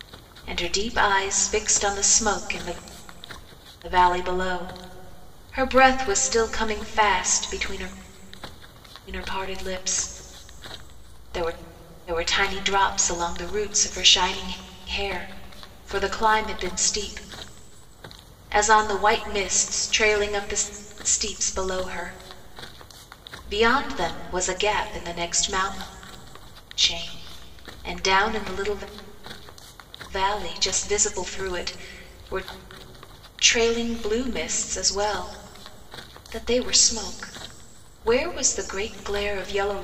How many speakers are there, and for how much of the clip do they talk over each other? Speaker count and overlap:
1, no overlap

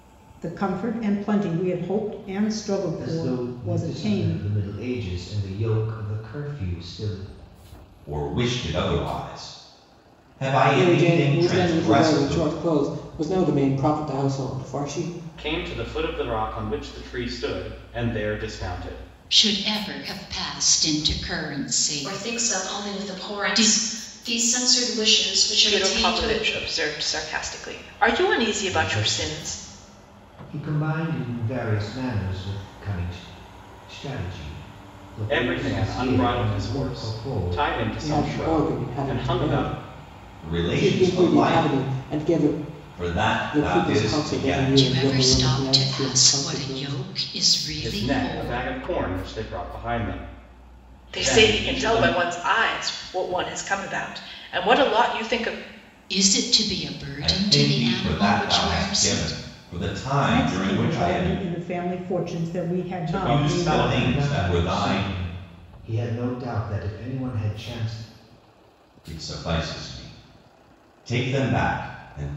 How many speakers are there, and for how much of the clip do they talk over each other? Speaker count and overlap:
8, about 33%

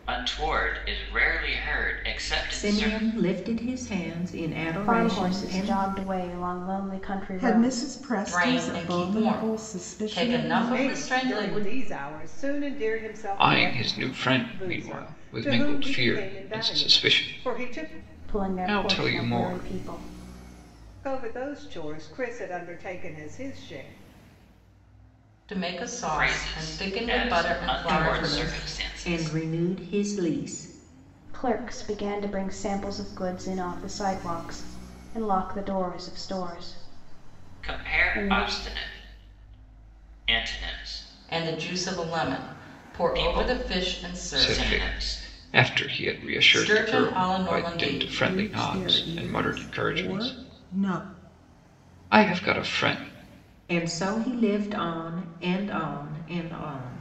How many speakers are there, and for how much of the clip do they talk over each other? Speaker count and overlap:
7, about 37%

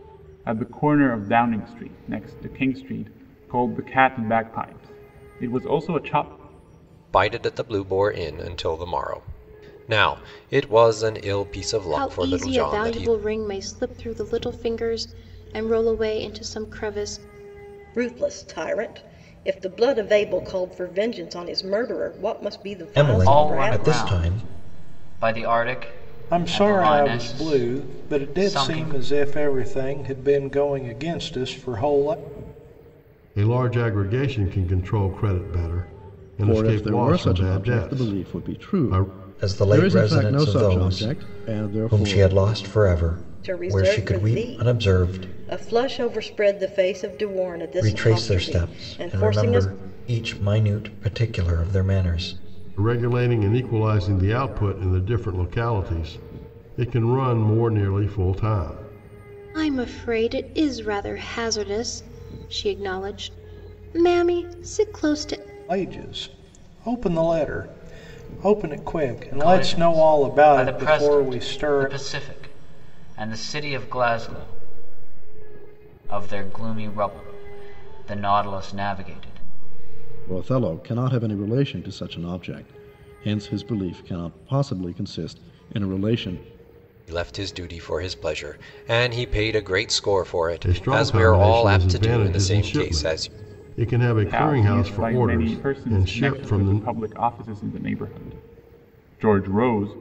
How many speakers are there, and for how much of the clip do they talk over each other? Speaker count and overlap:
9, about 23%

